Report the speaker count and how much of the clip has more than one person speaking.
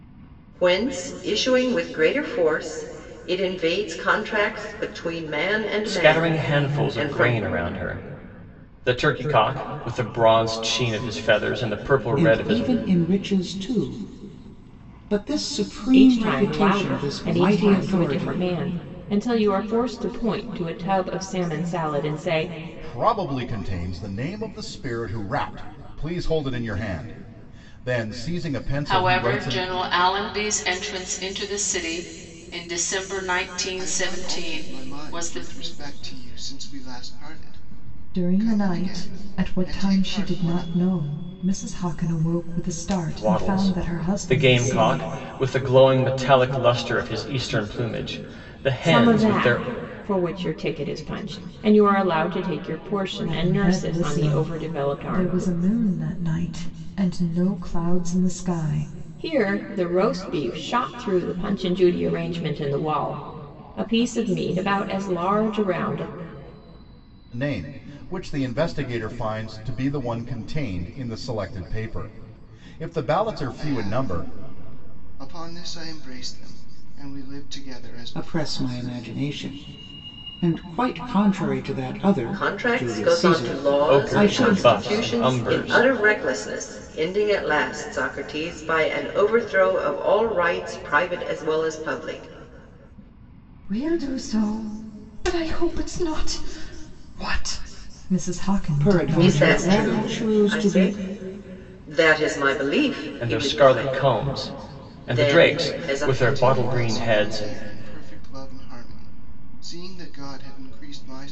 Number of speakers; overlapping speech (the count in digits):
8, about 23%